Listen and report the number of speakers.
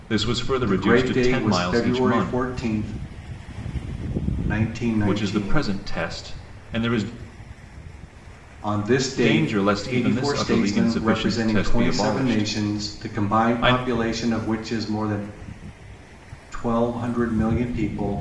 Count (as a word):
two